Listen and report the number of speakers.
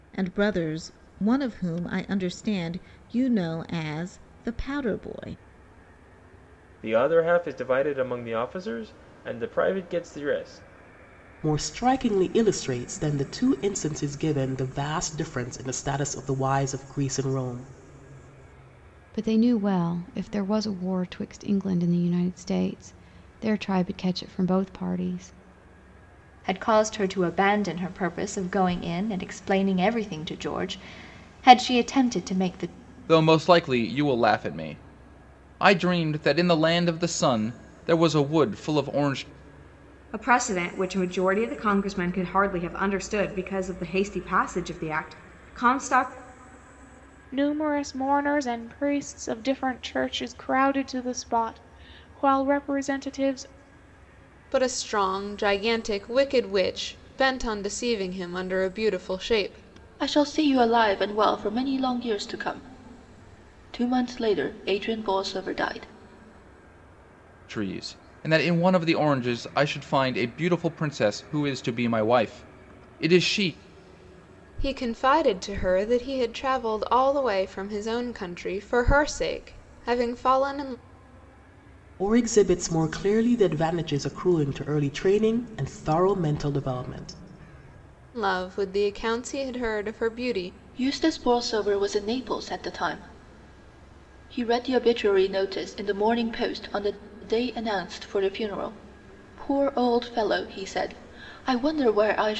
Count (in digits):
10